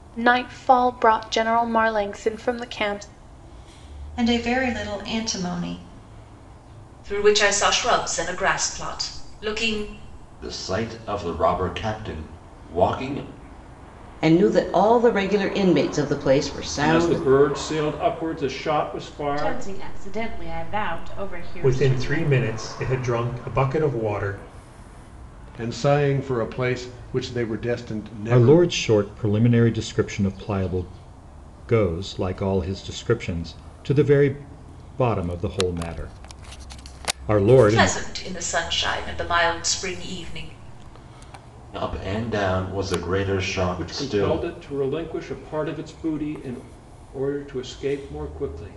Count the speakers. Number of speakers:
10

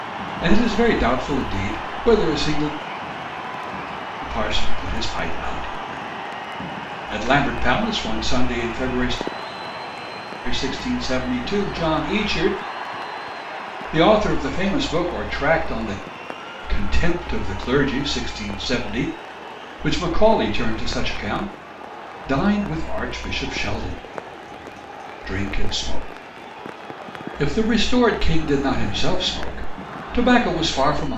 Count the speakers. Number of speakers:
1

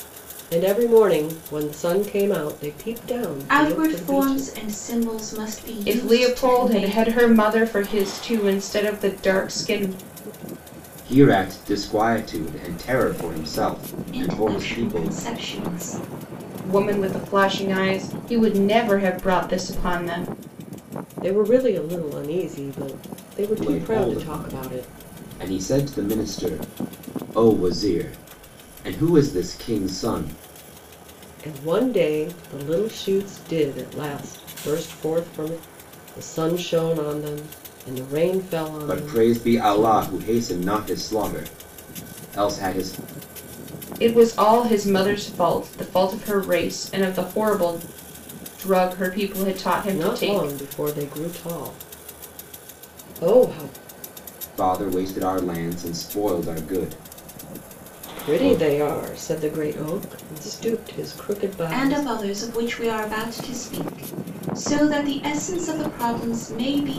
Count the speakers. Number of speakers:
4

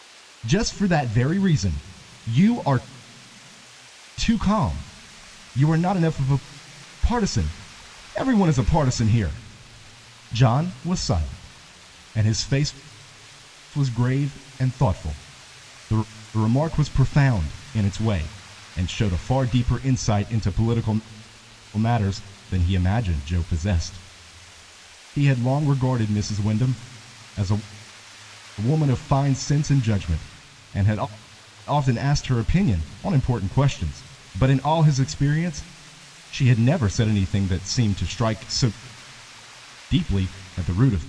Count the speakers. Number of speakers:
1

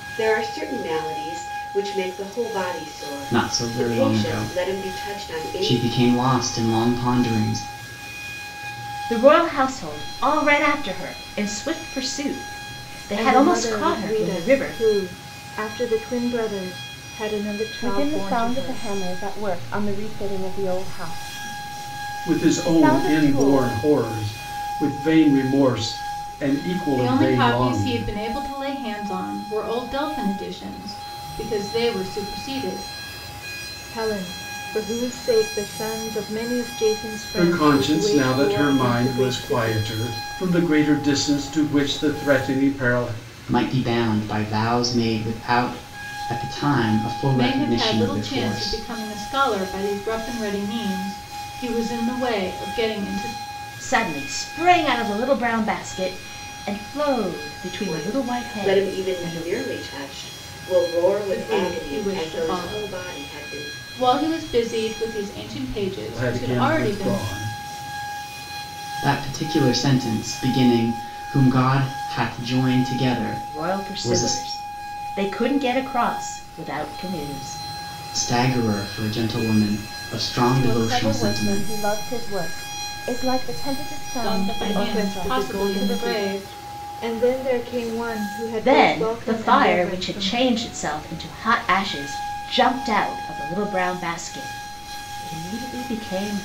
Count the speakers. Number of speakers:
7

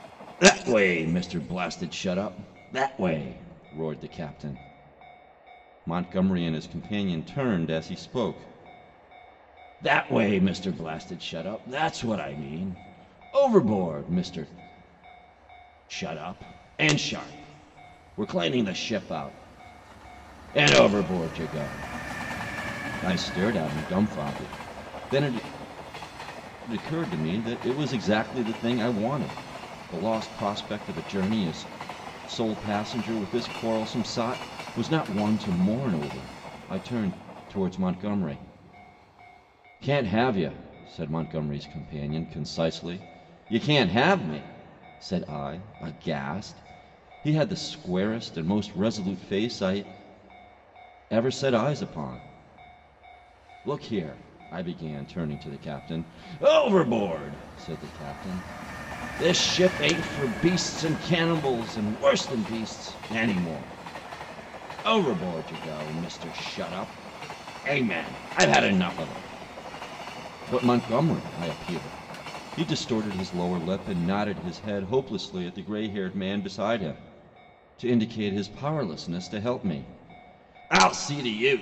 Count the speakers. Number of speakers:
1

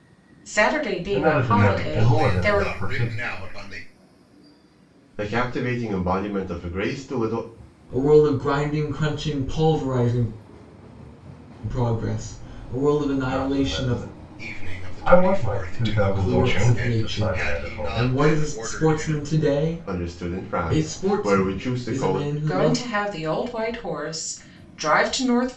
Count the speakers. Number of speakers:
5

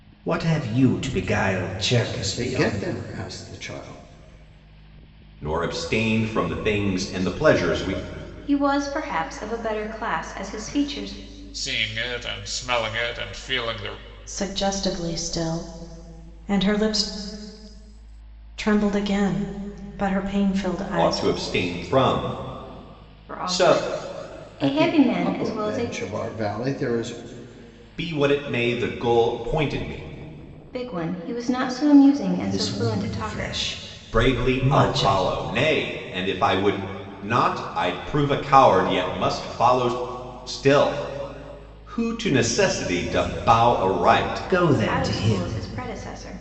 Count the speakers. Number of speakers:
6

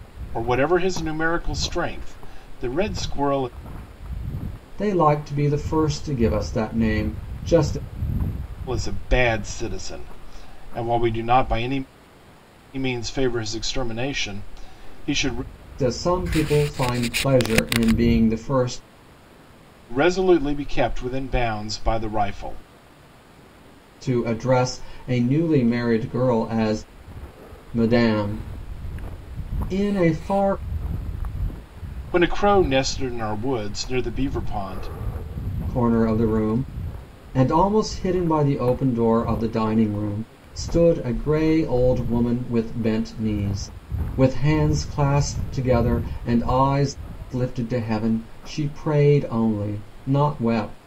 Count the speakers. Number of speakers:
2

